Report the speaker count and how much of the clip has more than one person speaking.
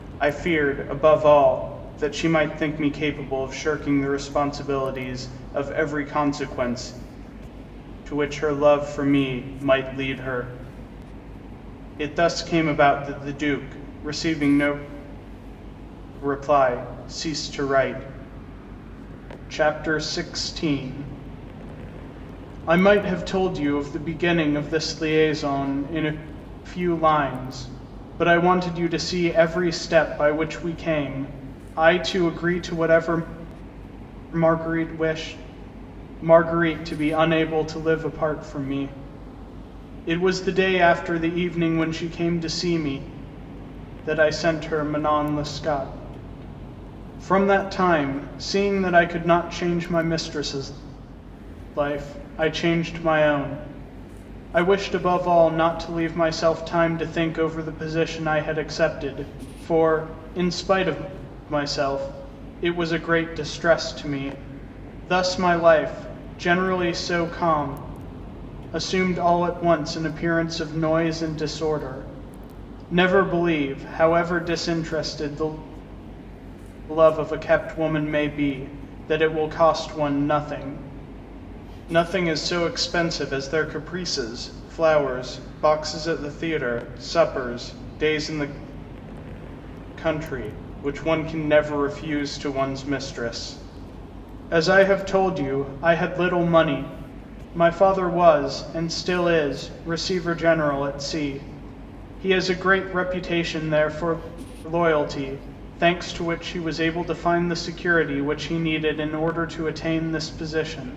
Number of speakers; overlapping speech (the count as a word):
one, no overlap